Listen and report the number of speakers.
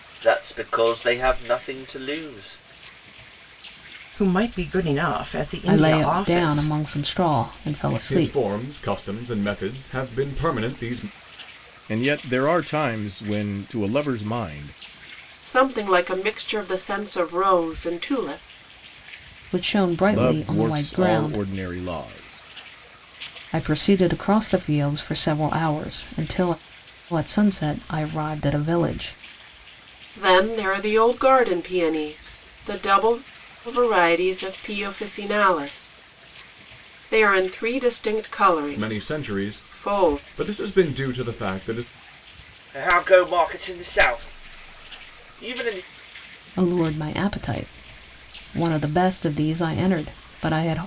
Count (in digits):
6